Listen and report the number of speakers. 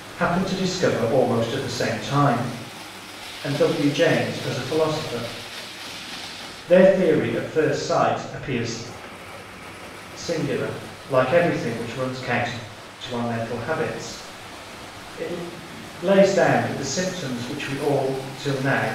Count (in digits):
1